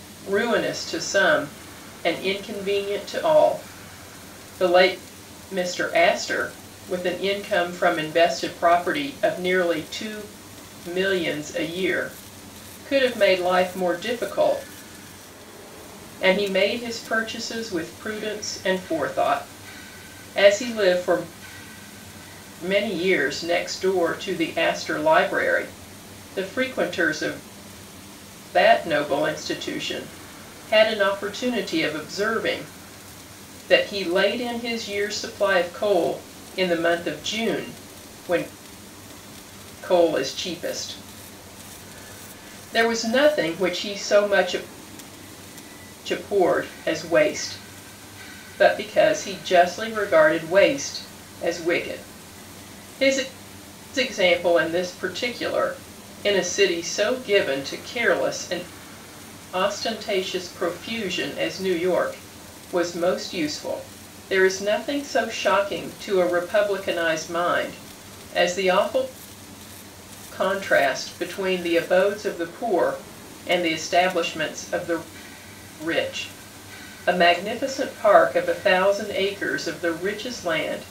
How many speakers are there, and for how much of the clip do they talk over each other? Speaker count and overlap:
one, no overlap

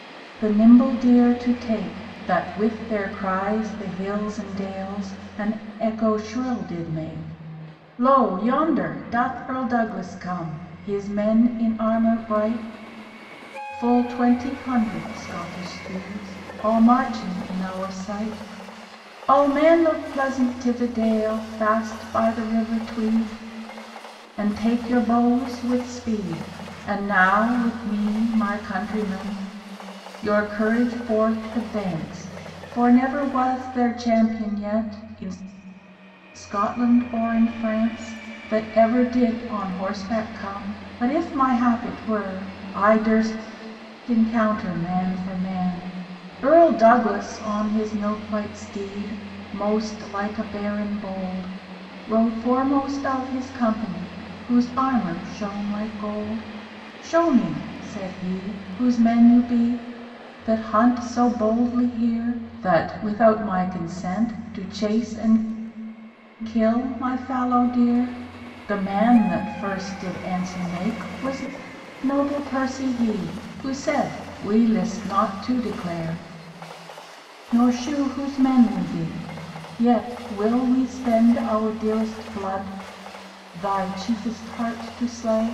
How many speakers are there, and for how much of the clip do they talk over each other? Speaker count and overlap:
one, no overlap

